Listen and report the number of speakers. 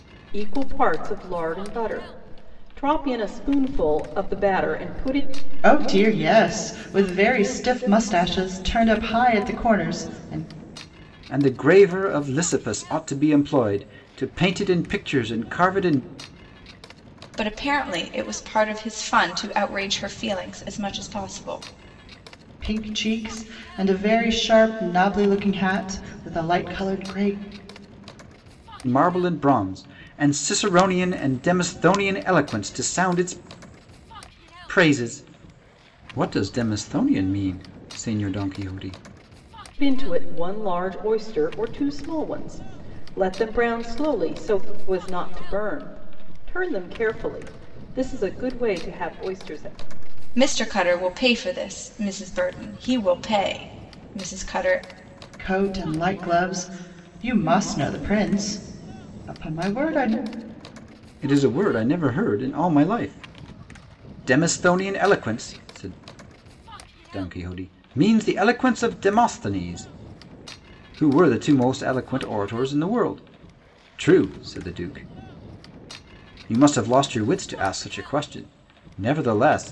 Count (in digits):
4